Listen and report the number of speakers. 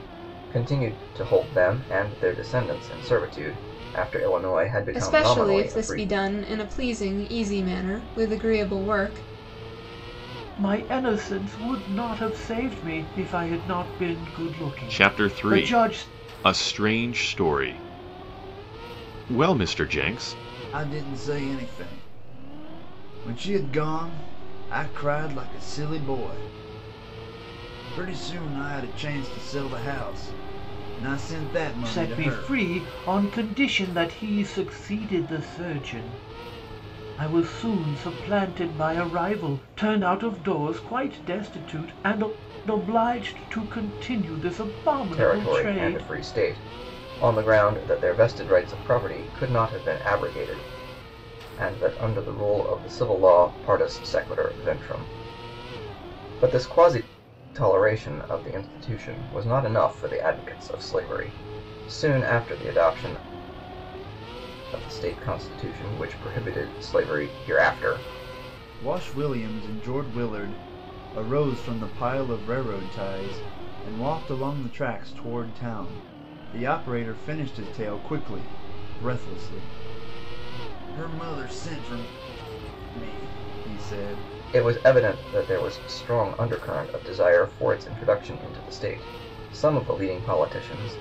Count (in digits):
5